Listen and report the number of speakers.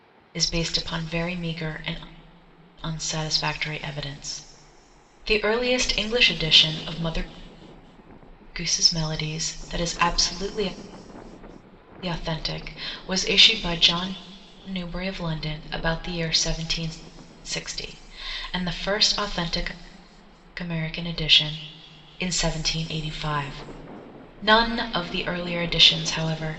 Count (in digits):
1